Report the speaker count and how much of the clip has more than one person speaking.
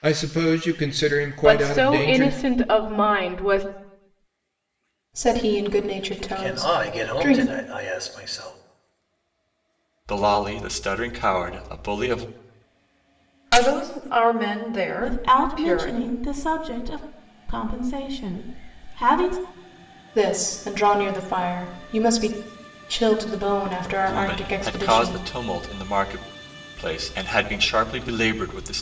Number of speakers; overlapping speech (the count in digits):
7, about 15%